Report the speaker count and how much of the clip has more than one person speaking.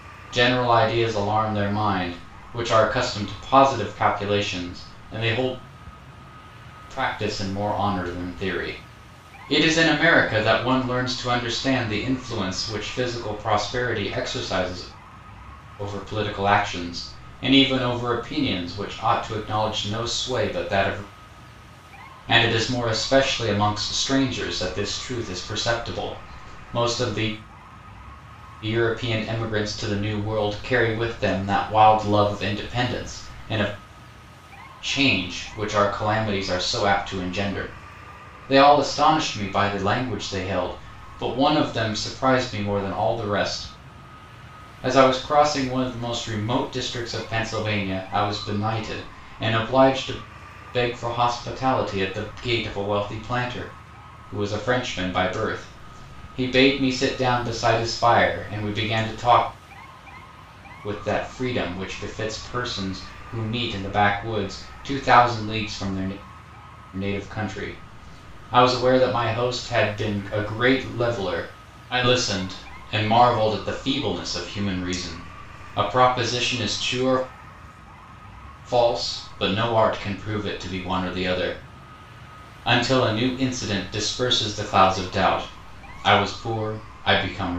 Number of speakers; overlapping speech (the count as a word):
one, no overlap